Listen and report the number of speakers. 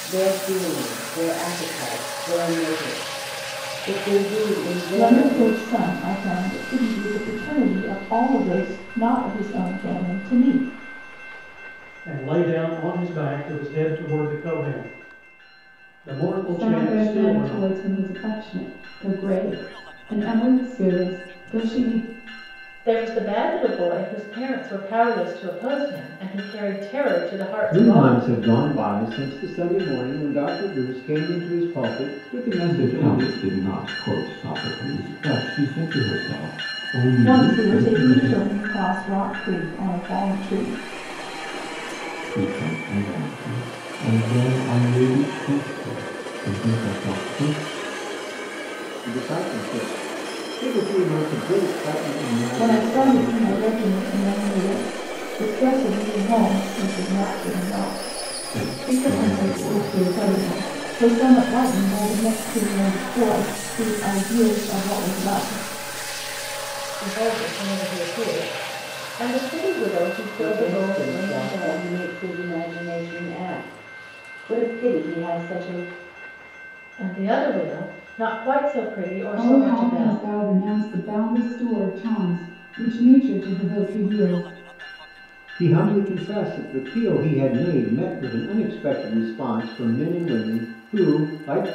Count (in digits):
7